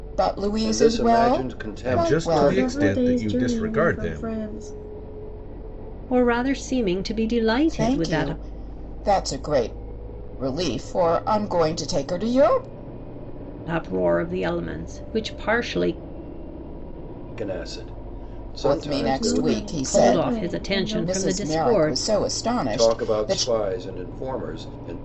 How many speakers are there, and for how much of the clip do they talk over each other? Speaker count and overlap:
five, about 34%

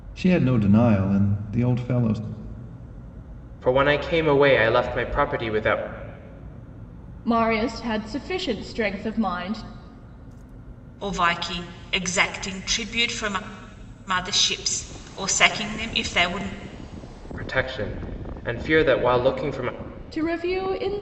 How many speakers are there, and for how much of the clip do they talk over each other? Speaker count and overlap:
four, no overlap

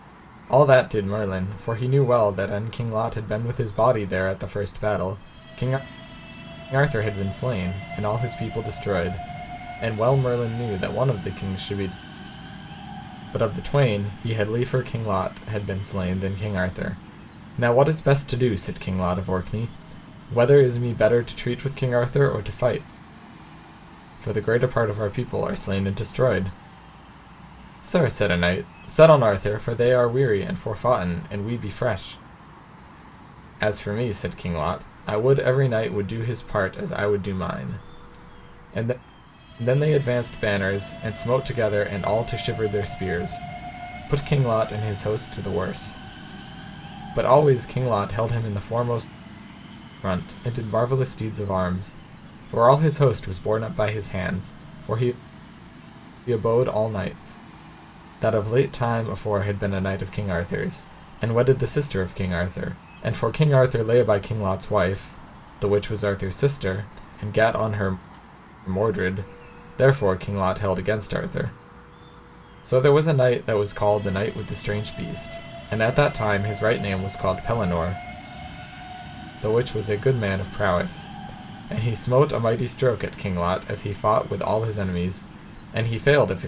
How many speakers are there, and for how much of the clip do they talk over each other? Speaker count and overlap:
one, no overlap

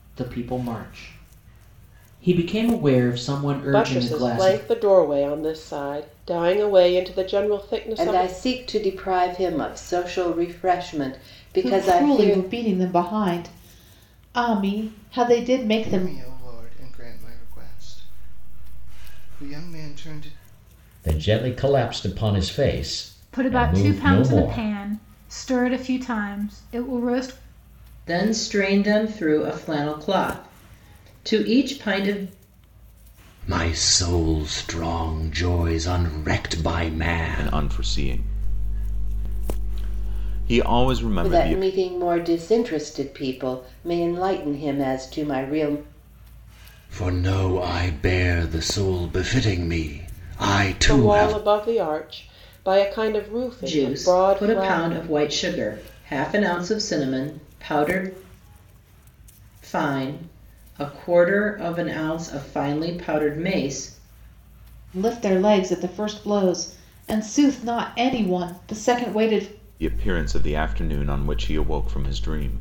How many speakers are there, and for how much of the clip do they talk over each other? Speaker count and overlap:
ten, about 9%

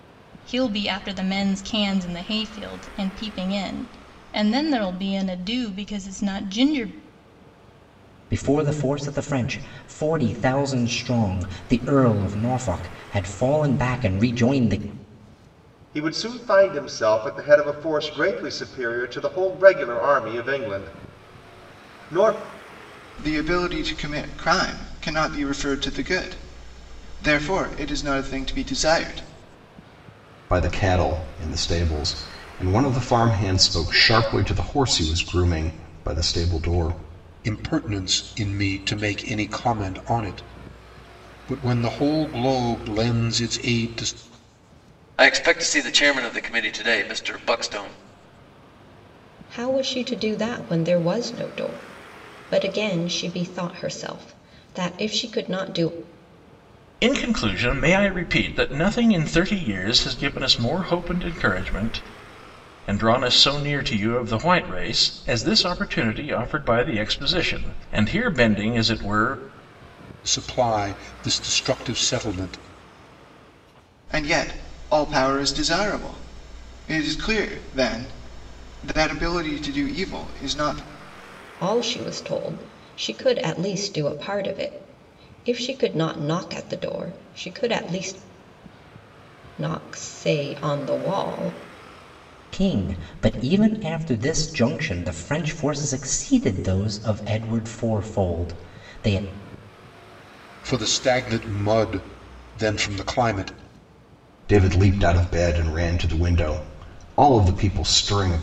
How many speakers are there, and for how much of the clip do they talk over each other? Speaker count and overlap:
nine, no overlap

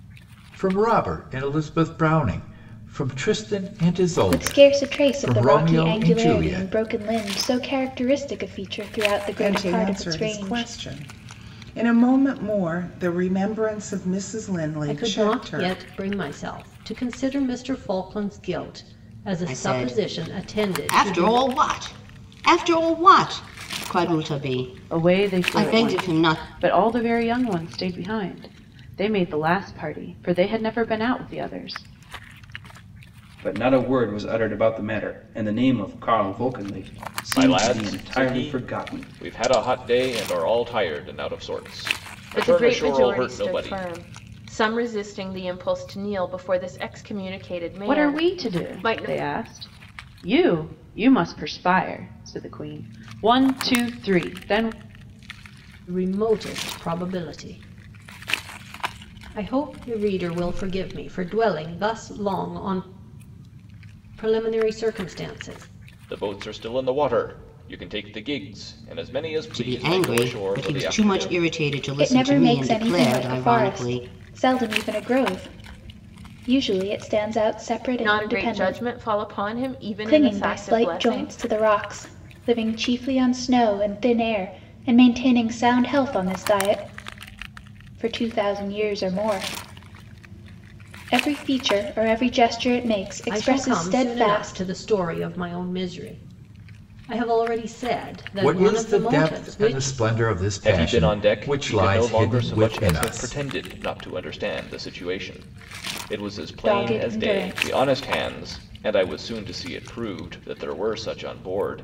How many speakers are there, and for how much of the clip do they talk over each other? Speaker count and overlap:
nine, about 23%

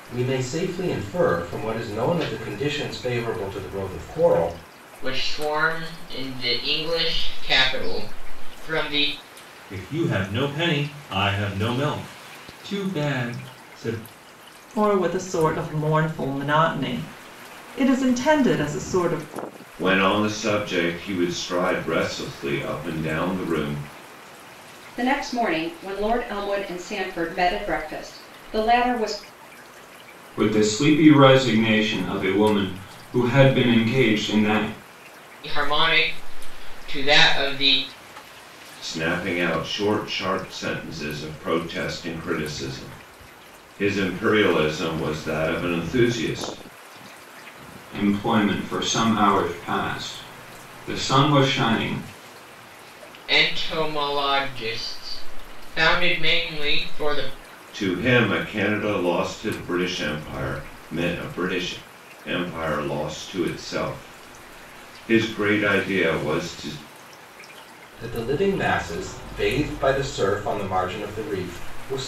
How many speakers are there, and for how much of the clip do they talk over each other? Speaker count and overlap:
seven, no overlap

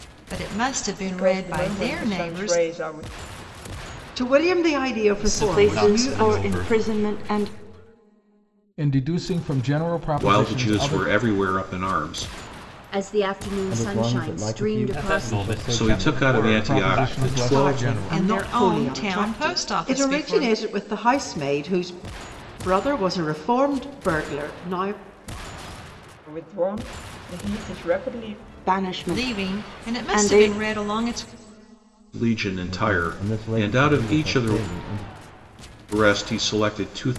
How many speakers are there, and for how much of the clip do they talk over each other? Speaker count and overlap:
nine, about 39%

